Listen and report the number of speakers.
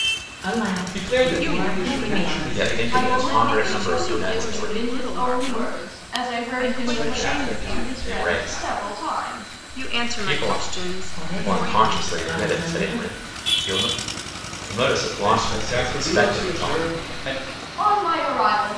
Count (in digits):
5